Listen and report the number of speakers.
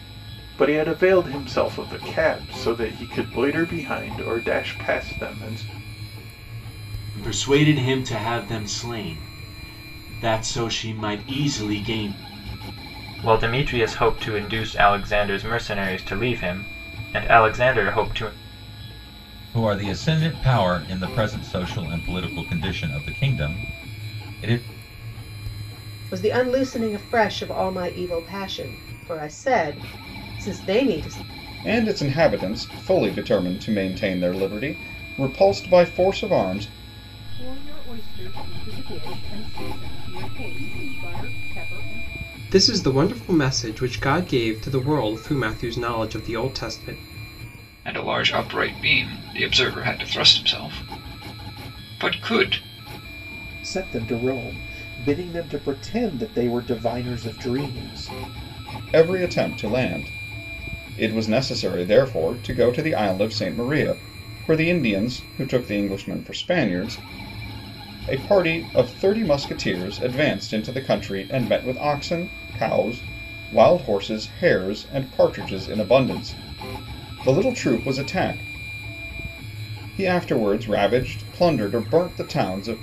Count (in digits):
10